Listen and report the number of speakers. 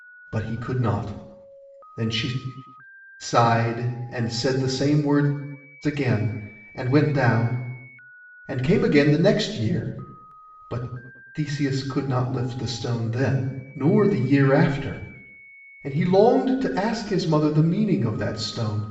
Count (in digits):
1